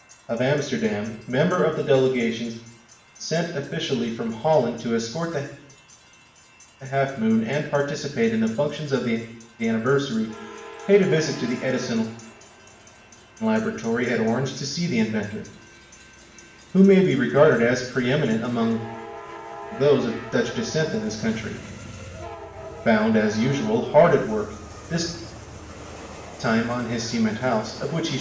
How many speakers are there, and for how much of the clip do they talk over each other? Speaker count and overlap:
one, no overlap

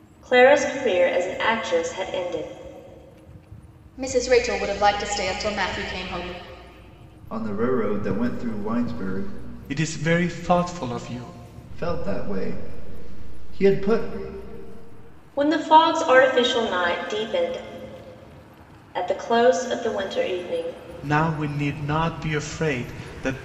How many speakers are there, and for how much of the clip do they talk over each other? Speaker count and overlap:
four, no overlap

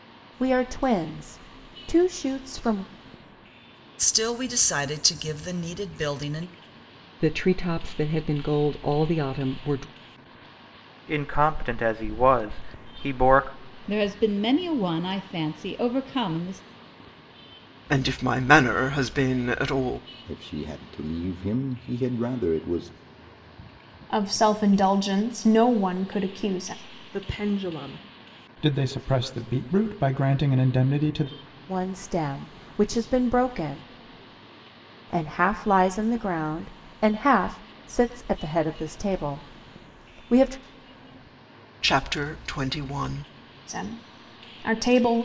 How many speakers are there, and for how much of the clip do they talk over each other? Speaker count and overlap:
ten, no overlap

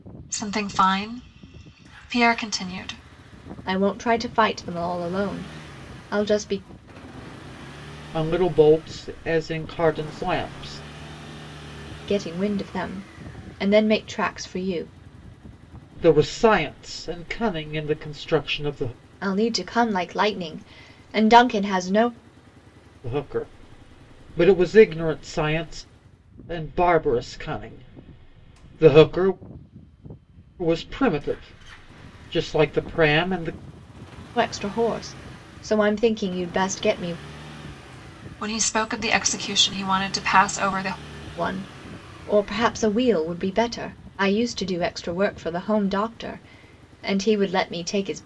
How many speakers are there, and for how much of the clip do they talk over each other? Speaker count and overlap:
three, no overlap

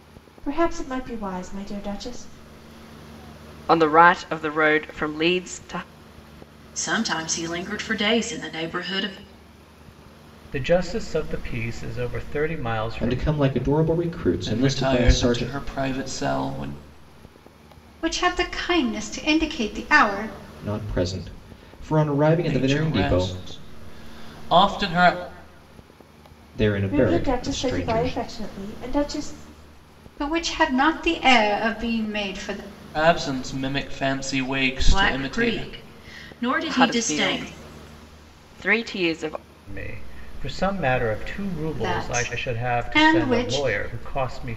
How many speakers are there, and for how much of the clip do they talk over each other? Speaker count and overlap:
seven, about 17%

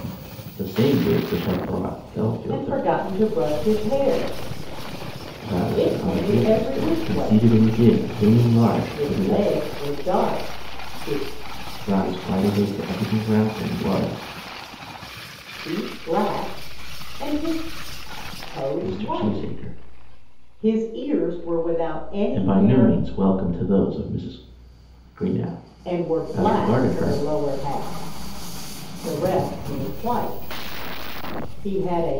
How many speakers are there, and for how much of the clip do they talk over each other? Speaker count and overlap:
two, about 17%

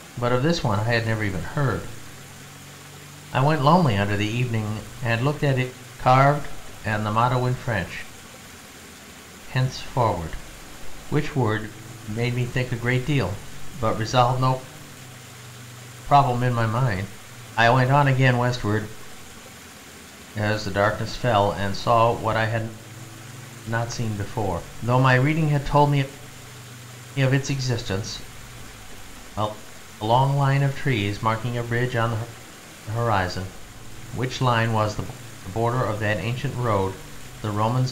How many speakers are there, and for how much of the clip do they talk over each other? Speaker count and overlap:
one, no overlap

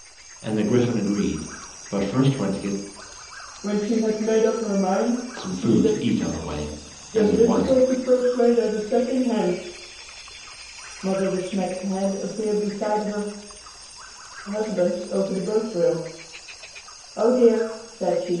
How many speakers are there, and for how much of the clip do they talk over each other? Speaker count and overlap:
two, about 7%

